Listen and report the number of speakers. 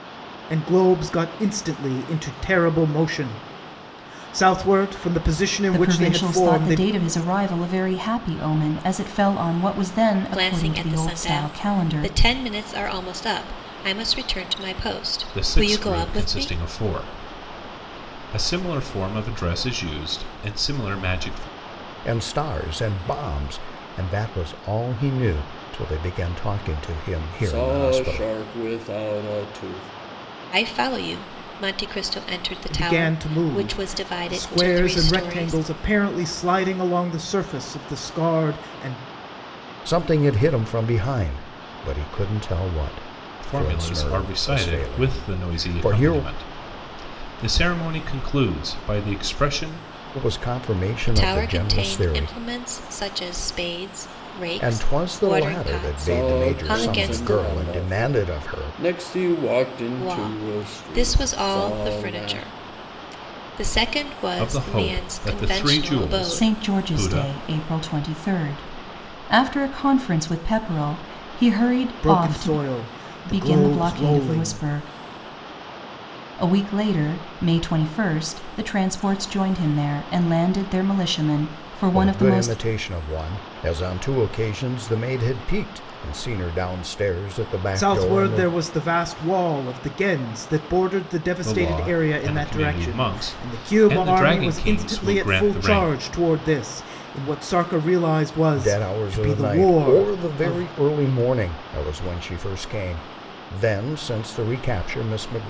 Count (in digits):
6